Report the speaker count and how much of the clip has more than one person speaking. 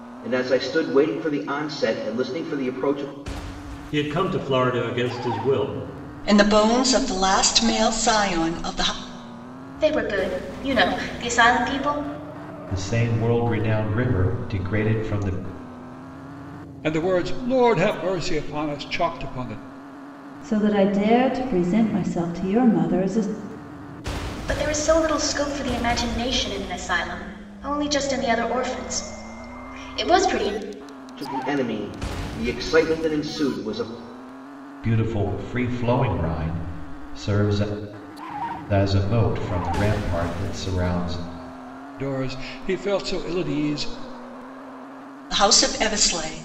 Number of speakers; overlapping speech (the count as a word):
seven, no overlap